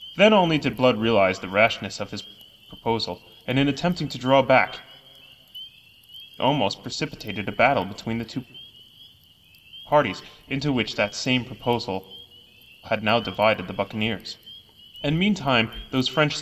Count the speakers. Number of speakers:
1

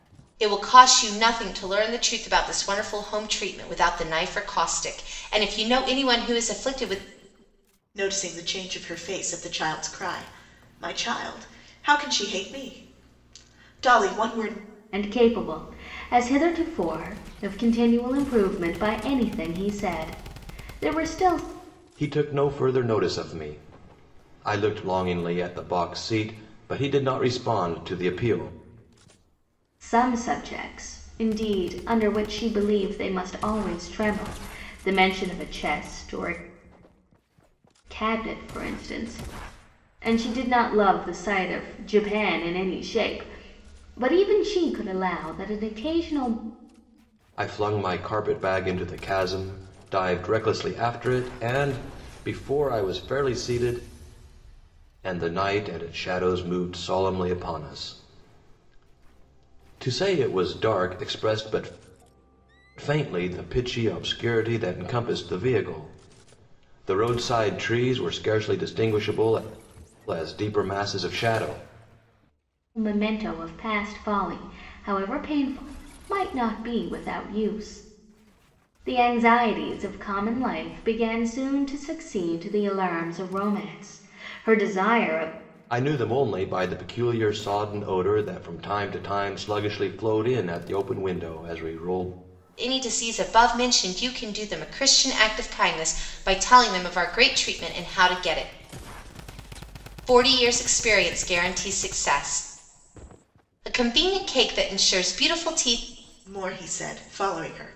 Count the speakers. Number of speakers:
4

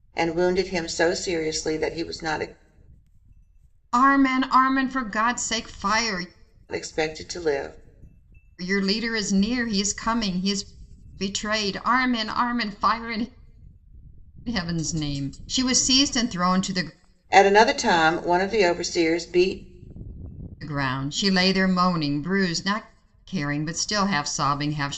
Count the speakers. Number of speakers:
2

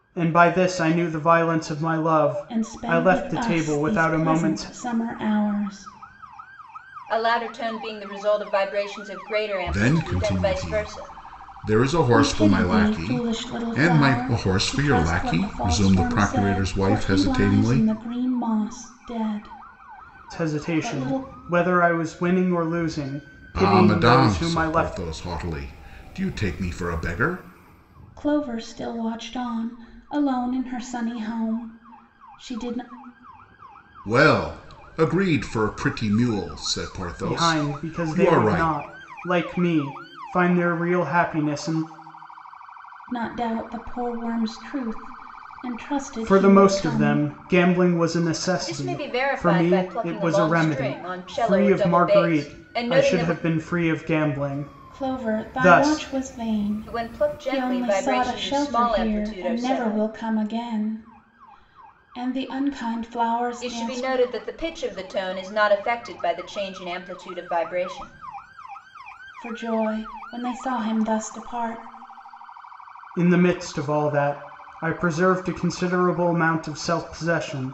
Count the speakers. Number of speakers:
4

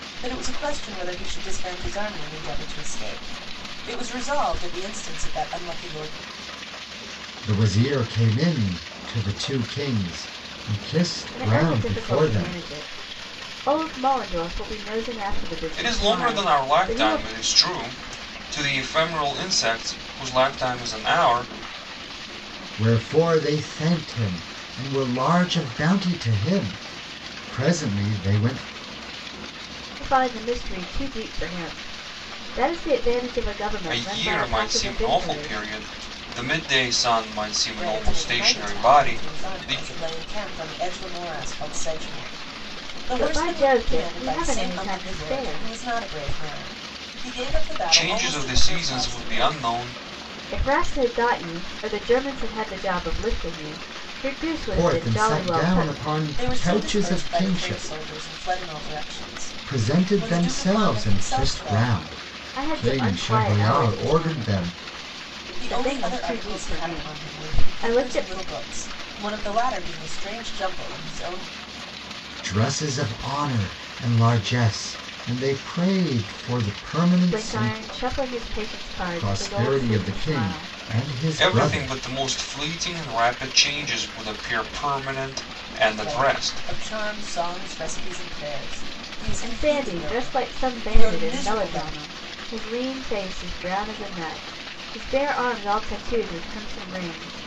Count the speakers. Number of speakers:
4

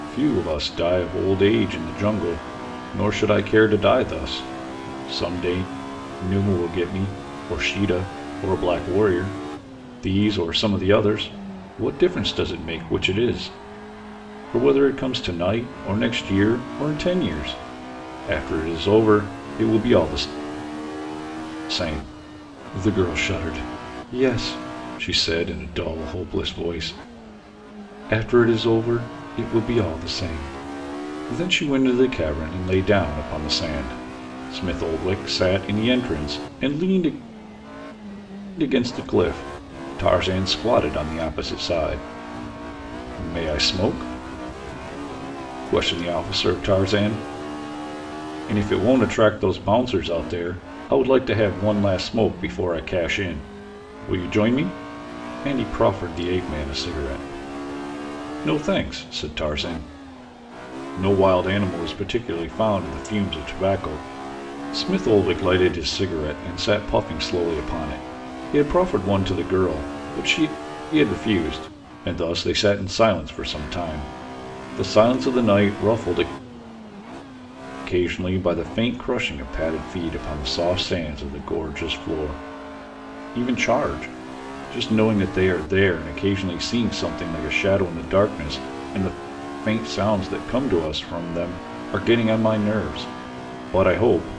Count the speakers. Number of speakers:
1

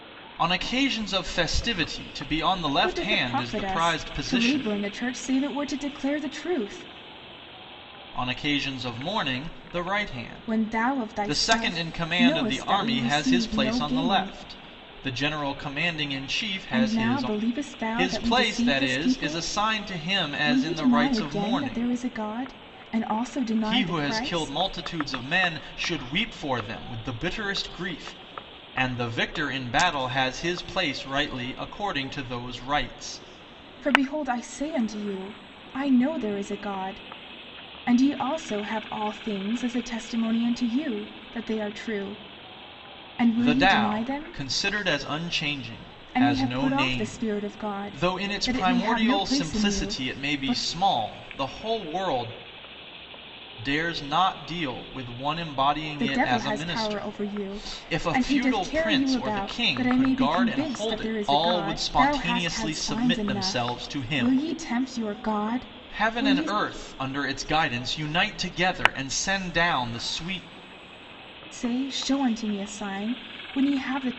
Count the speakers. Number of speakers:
2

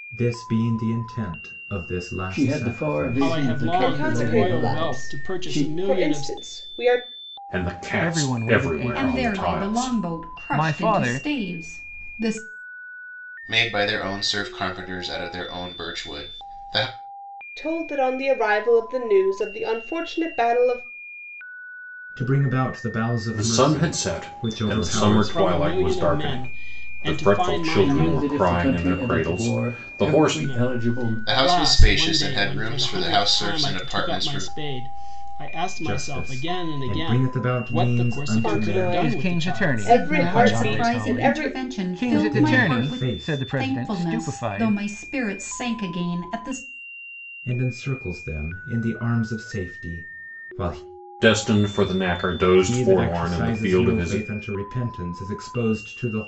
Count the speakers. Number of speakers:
8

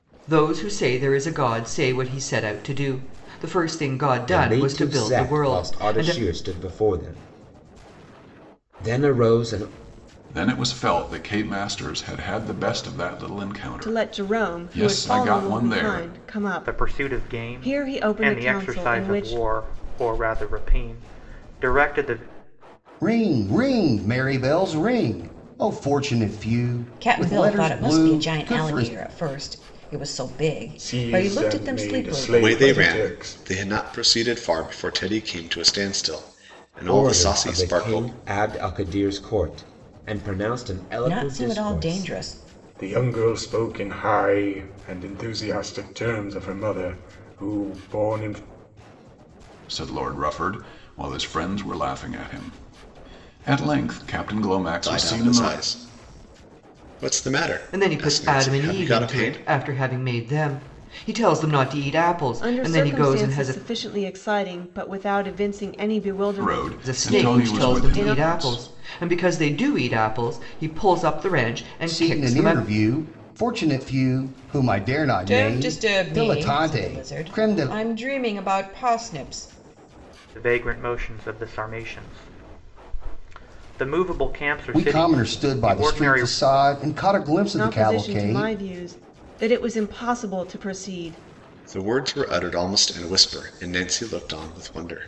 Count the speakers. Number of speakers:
9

